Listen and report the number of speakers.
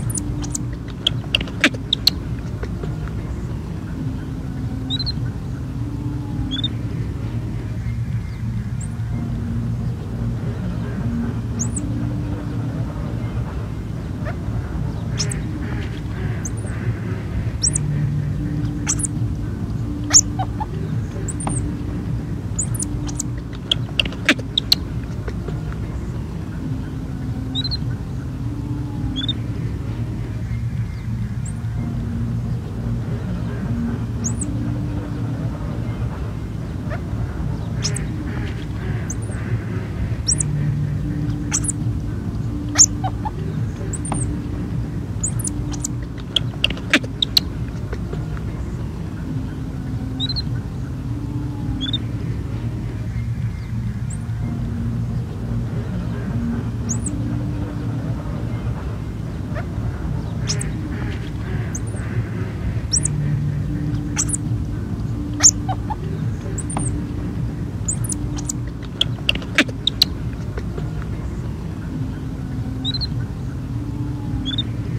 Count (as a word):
zero